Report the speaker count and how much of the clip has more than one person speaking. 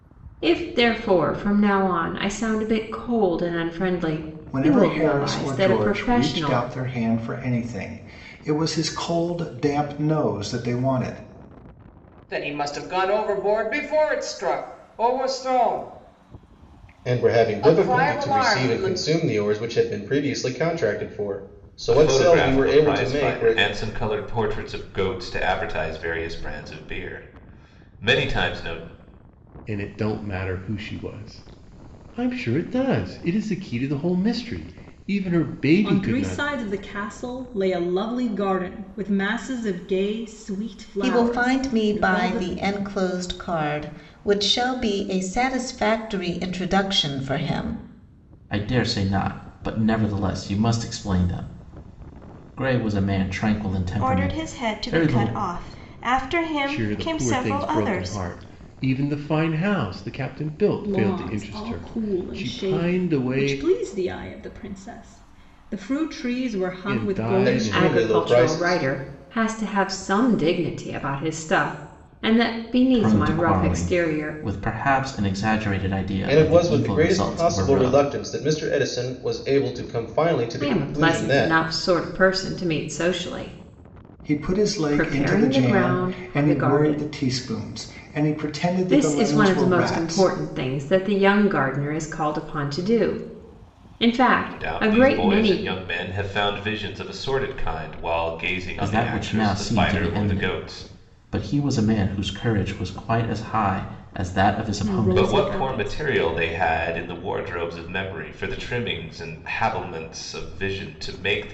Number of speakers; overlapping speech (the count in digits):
10, about 26%